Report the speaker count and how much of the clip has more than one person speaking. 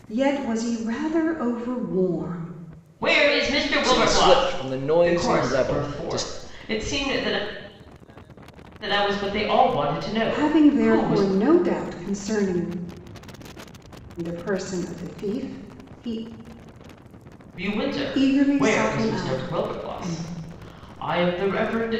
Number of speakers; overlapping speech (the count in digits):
3, about 24%